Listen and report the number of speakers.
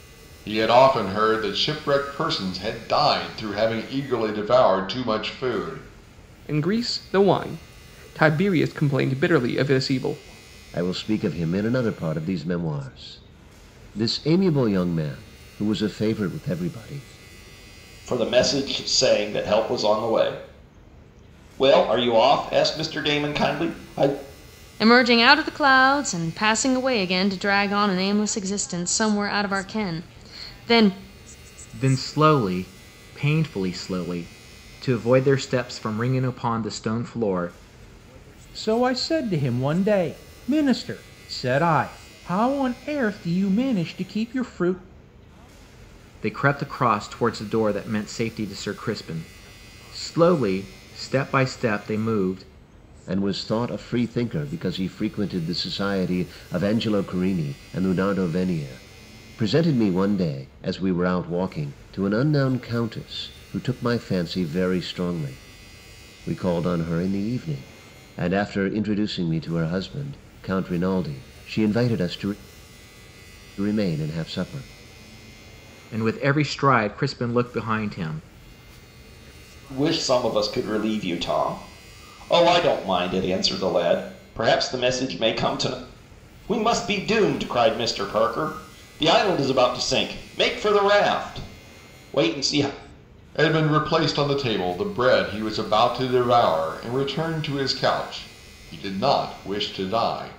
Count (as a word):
seven